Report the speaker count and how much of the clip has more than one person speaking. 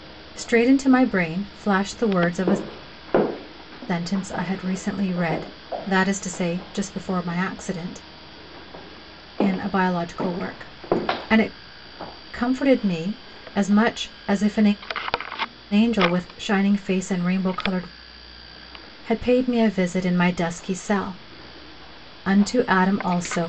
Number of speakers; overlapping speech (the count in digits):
1, no overlap